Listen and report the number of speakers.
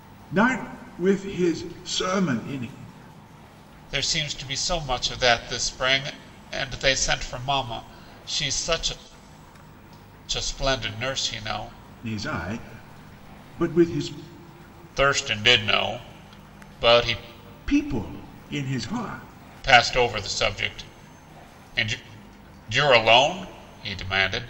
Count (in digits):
2